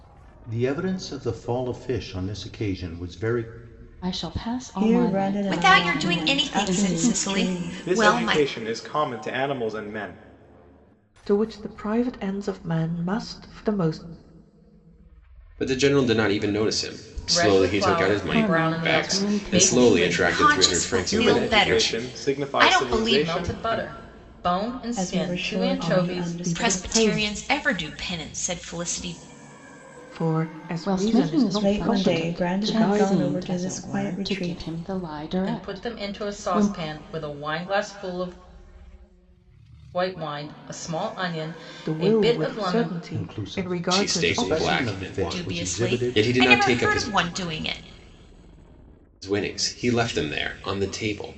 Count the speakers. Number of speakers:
8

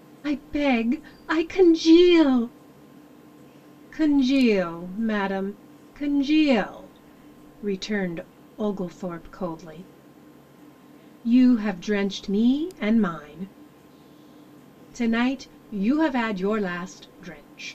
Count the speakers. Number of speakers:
1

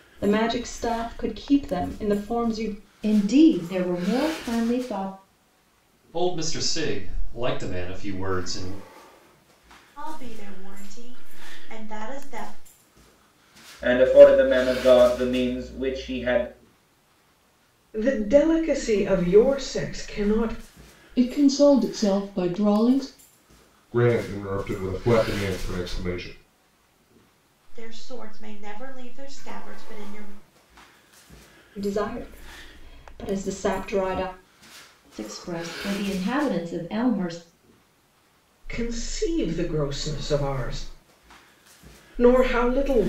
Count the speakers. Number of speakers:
8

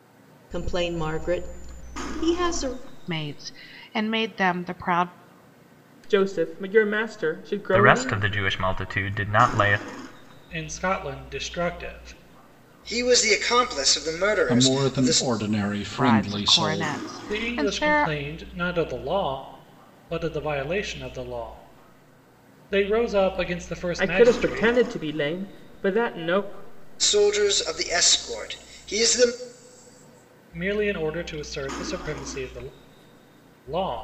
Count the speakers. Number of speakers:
7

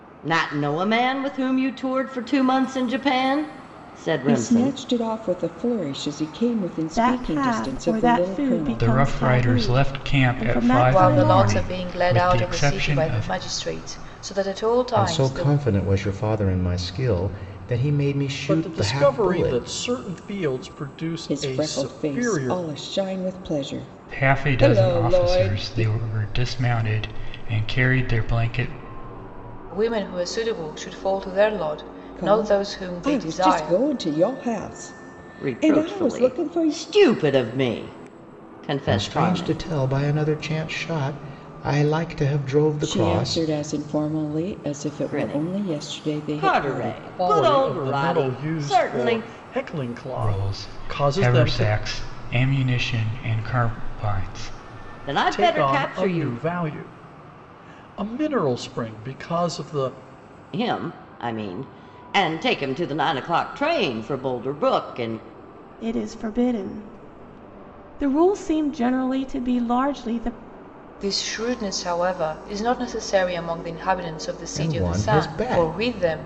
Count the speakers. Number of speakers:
7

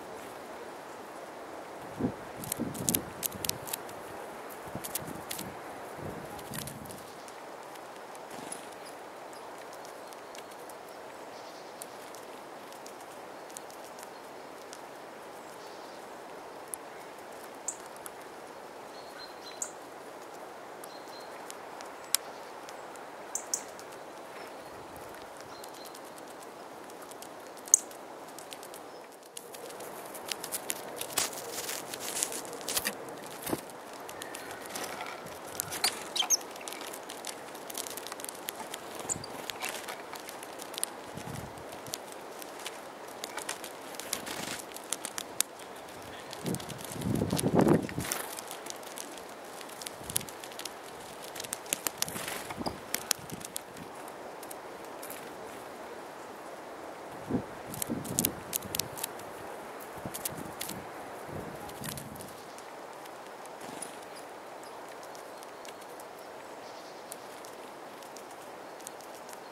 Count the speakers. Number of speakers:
0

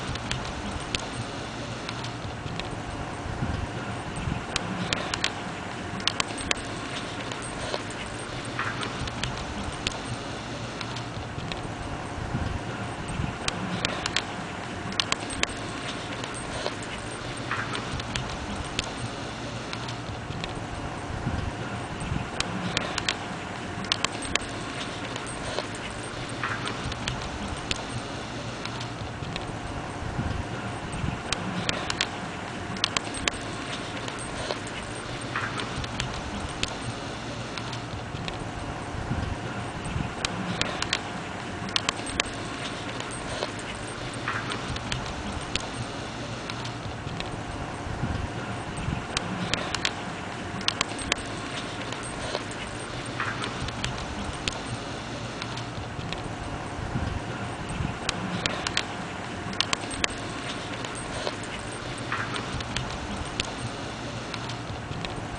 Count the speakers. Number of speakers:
0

